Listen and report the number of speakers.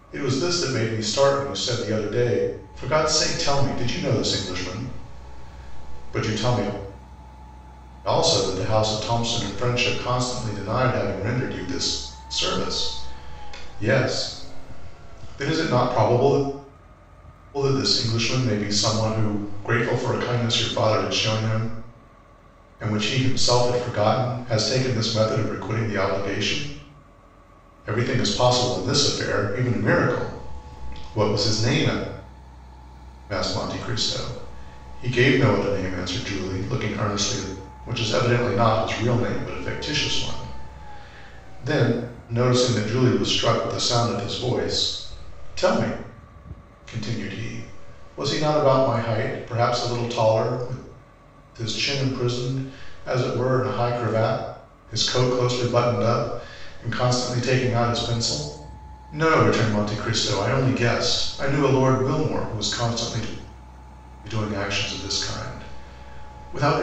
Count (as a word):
one